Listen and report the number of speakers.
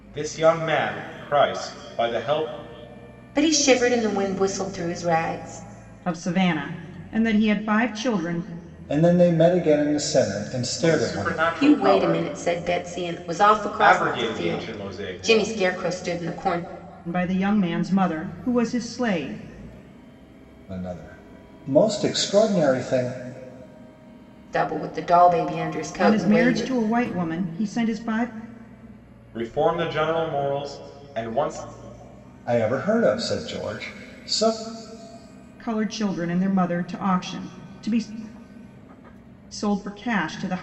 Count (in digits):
4